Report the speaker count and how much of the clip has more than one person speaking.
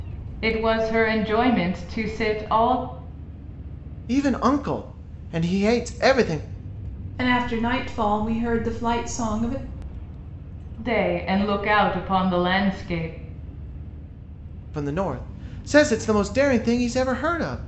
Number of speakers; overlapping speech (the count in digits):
3, no overlap